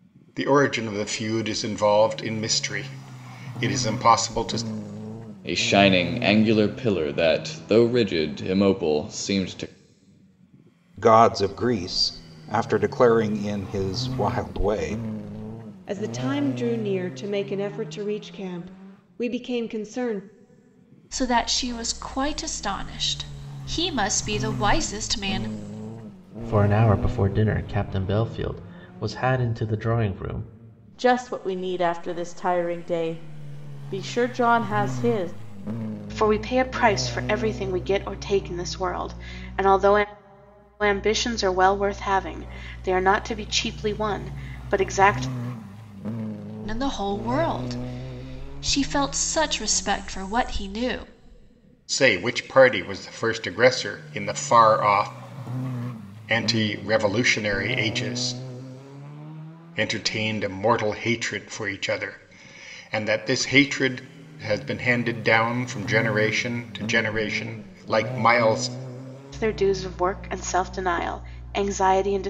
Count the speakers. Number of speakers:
8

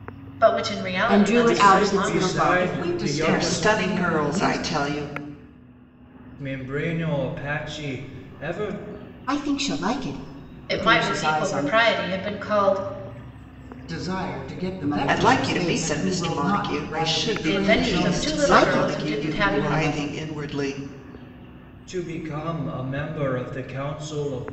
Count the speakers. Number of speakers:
5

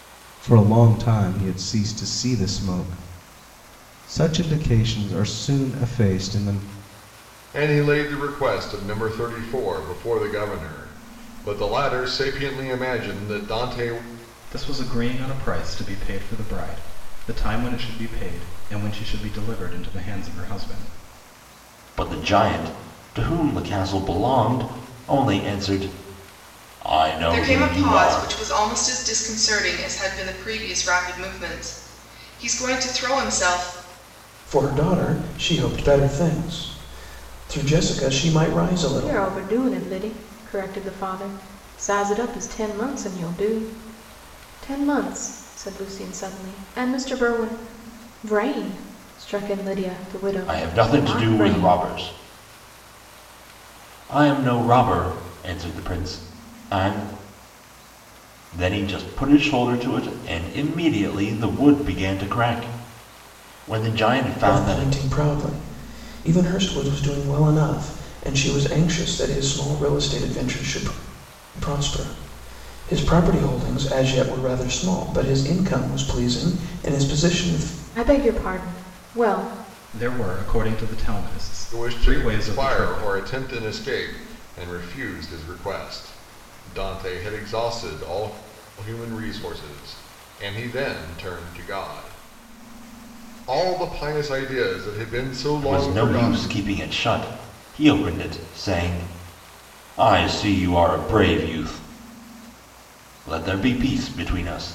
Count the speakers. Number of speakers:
7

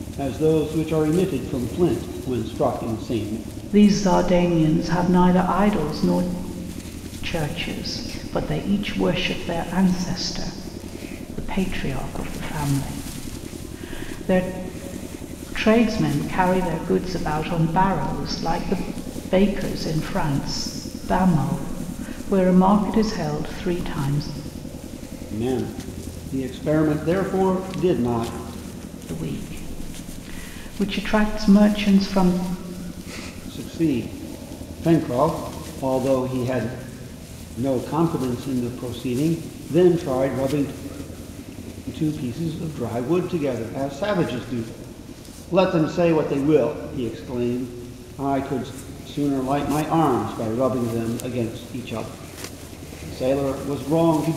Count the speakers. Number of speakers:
2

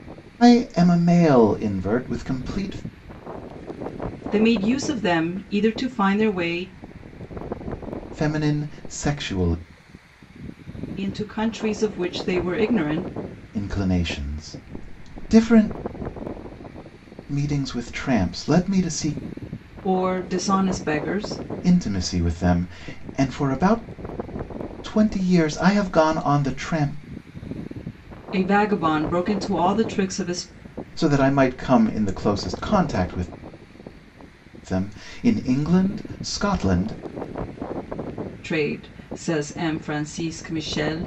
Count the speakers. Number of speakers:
2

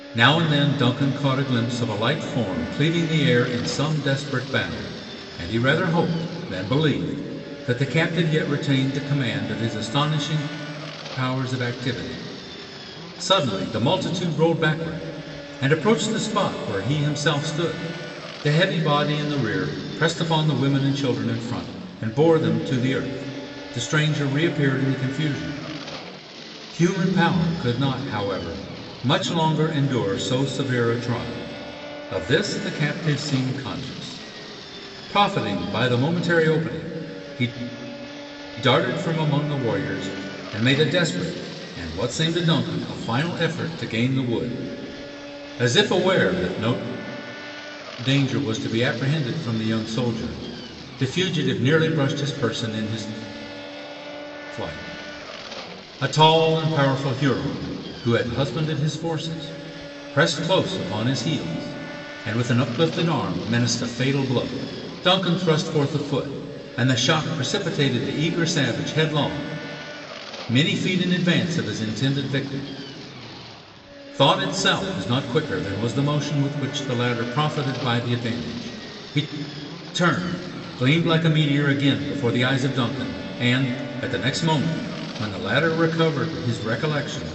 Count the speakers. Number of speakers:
1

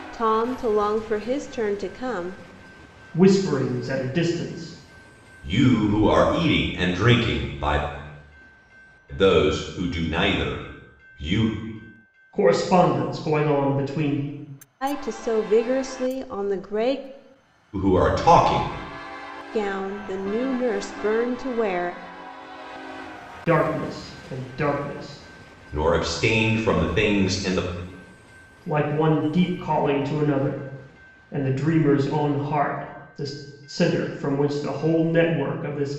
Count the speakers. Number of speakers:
3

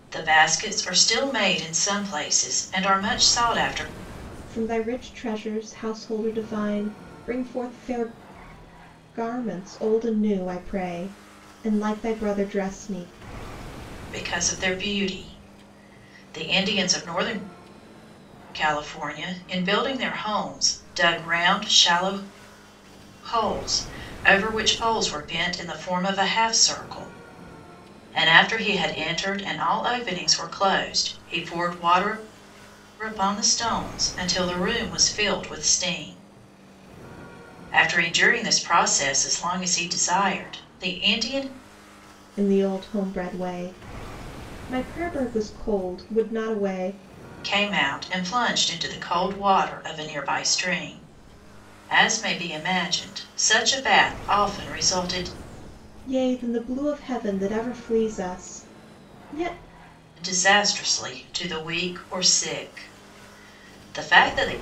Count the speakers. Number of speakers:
2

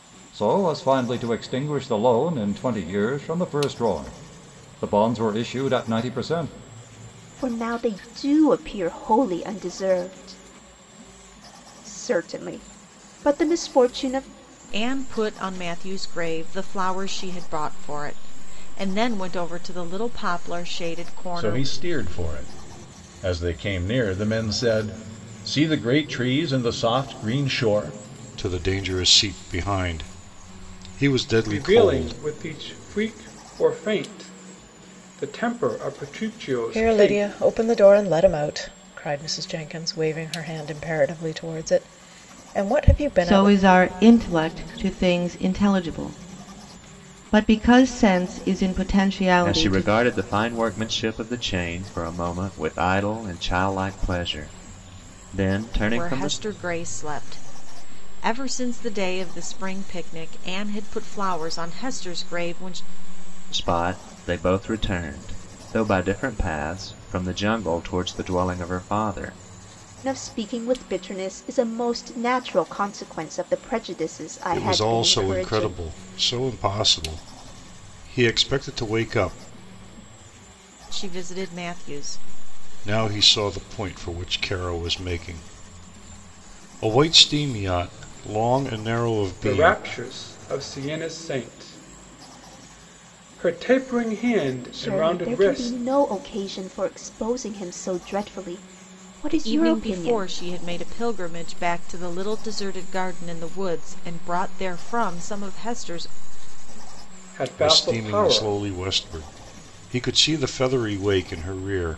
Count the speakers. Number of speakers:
9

